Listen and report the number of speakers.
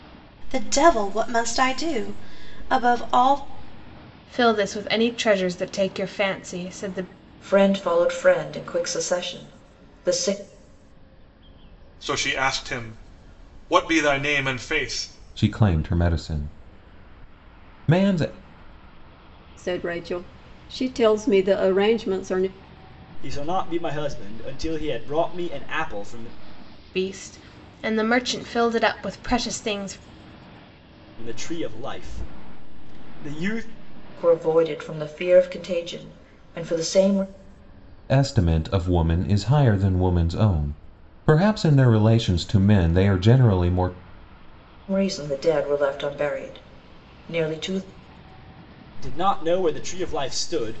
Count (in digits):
7